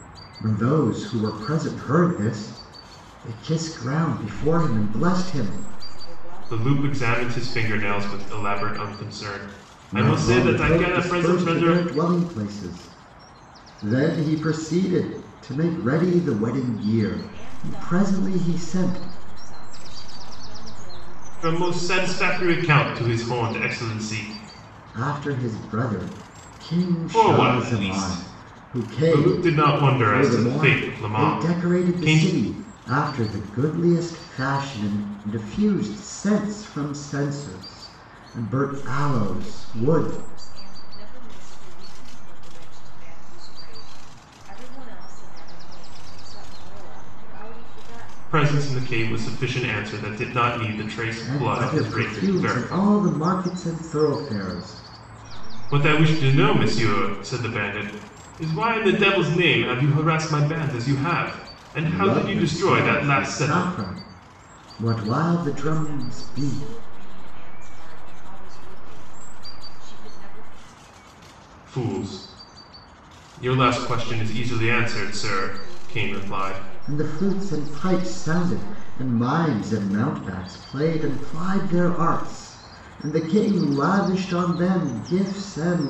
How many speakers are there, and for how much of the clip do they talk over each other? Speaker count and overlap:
3, about 34%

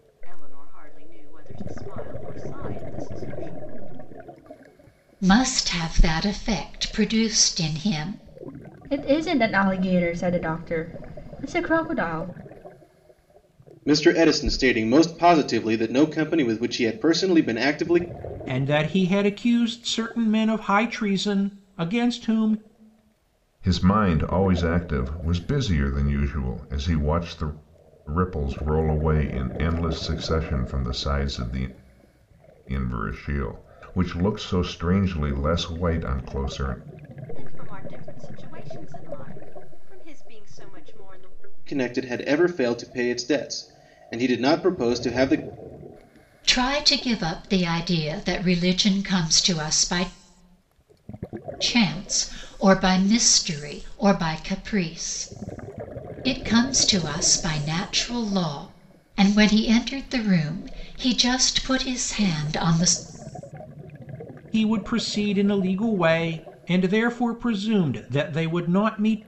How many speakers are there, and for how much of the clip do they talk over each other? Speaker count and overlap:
6, no overlap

